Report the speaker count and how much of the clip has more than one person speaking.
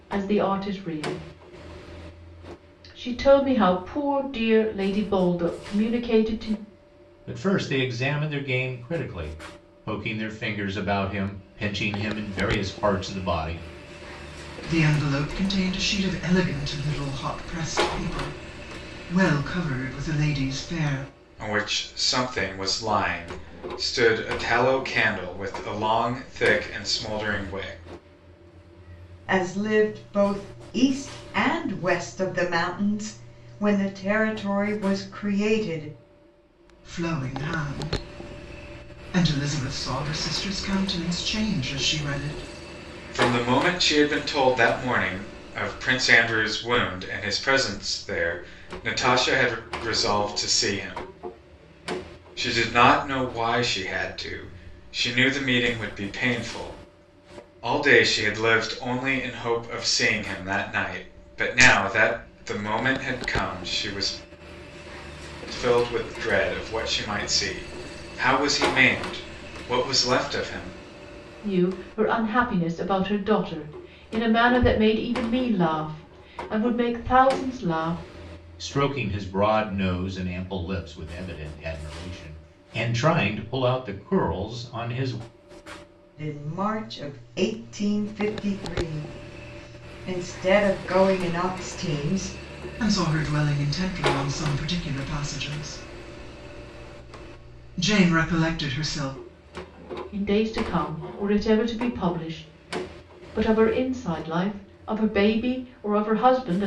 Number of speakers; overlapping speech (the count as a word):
five, no overlap